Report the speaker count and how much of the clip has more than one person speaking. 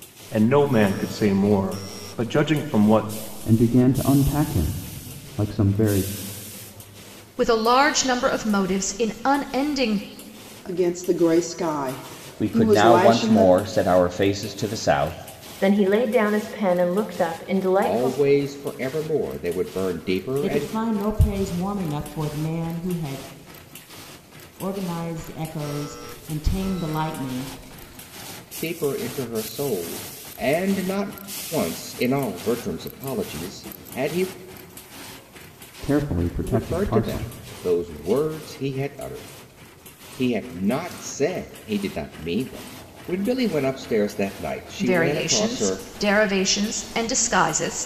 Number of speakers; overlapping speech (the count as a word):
eight, about 8%